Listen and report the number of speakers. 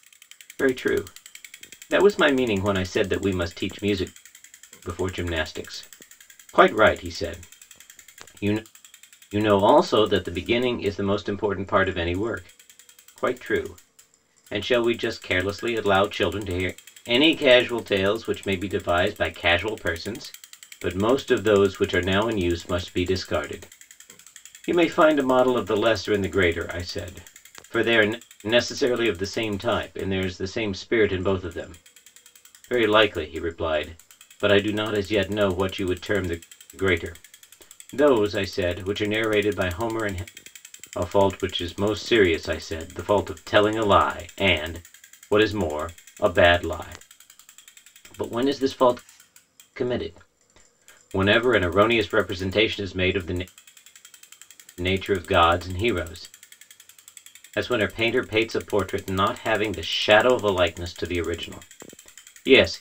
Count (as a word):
one